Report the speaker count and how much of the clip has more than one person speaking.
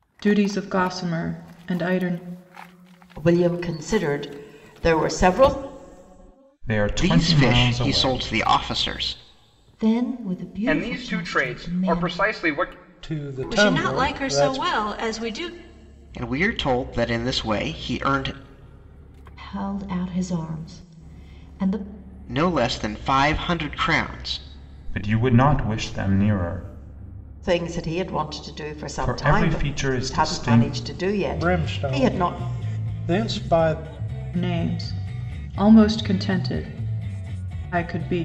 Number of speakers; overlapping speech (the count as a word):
eight, about 18%